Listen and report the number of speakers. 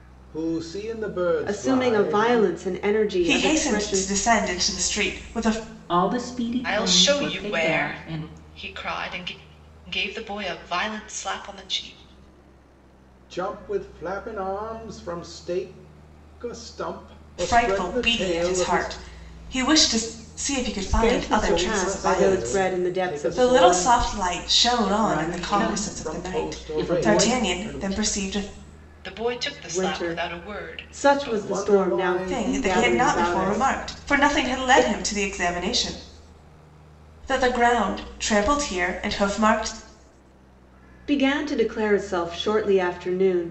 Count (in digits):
5